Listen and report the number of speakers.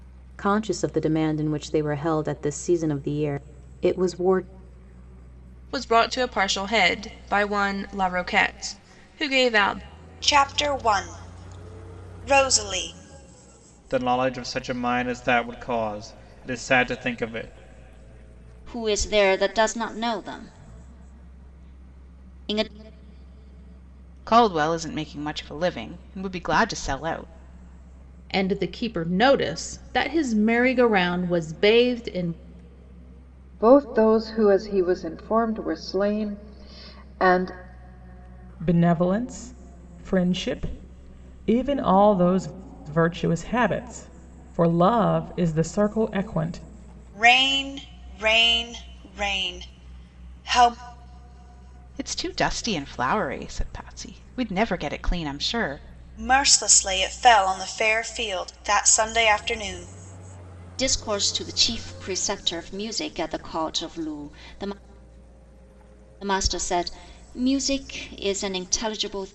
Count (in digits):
9